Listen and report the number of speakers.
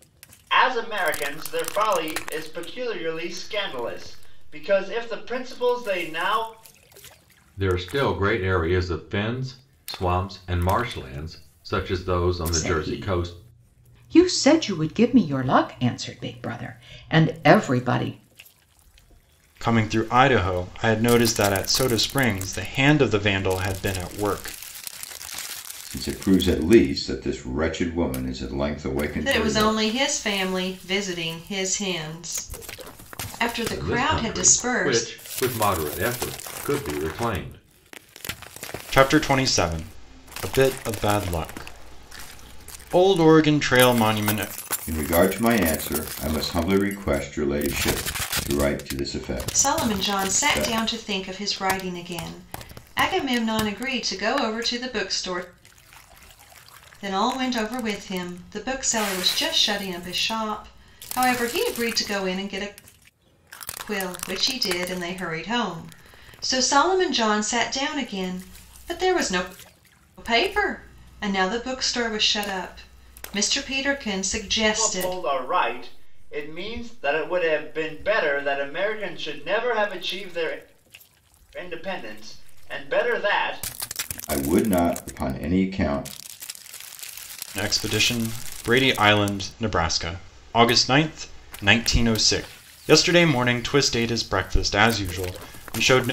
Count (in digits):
6